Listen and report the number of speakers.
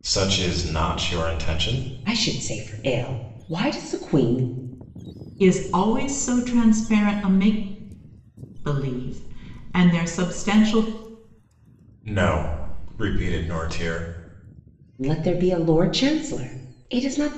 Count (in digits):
3